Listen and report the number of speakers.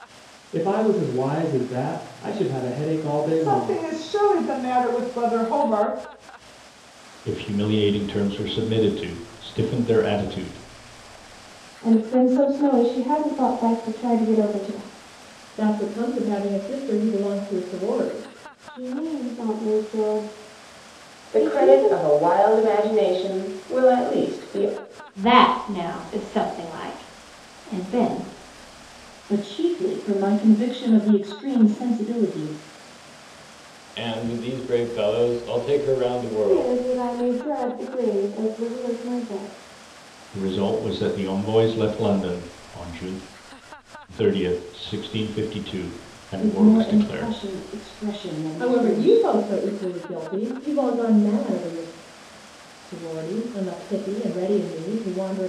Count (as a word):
ten